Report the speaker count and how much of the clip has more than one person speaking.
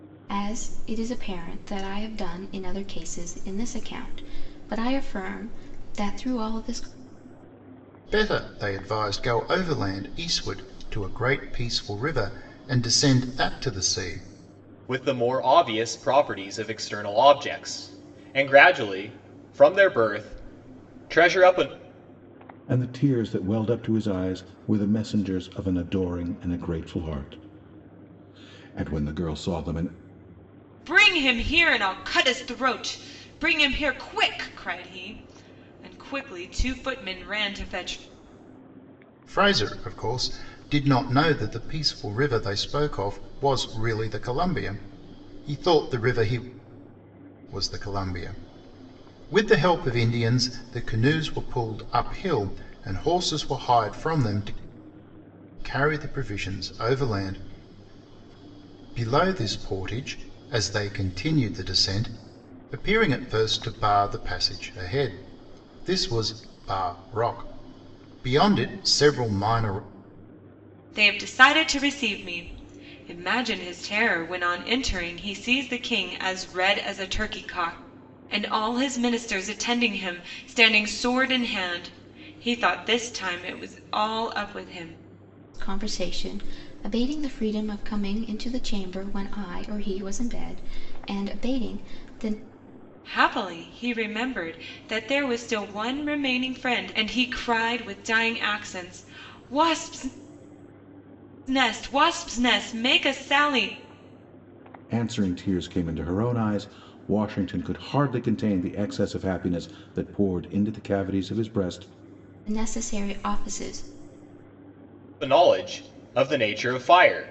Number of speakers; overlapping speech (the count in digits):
5, no overlap